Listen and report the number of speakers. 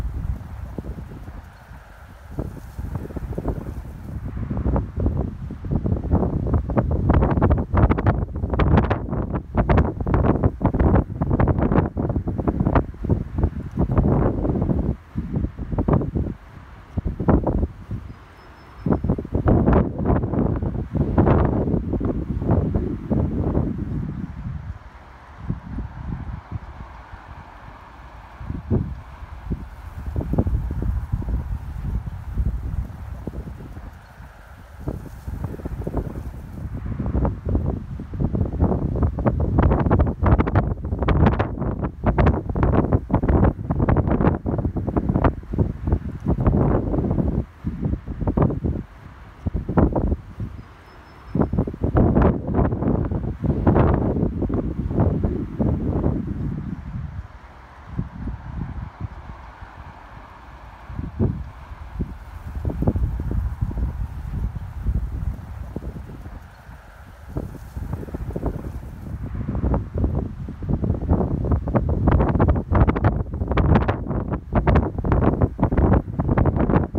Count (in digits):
0